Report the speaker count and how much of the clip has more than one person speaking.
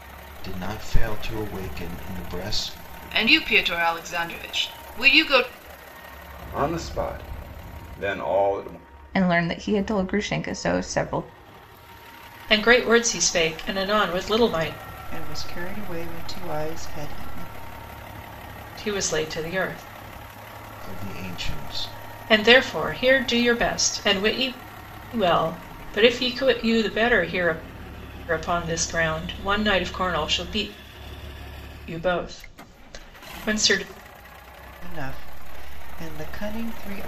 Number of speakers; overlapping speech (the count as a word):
six, no overlap